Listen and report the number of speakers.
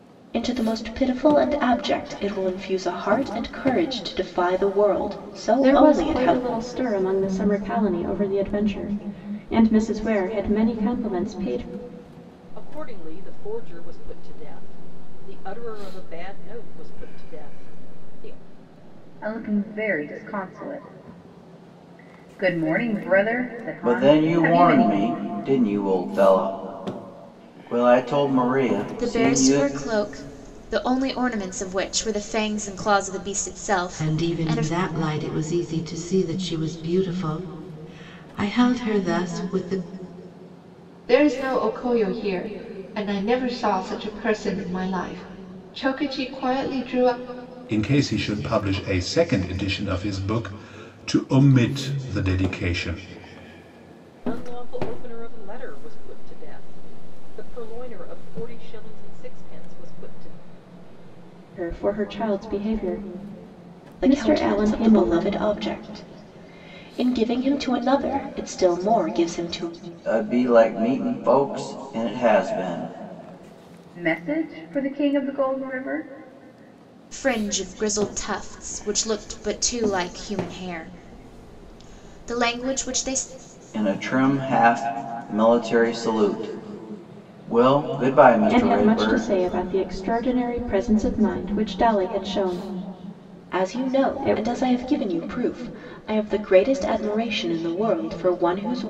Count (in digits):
9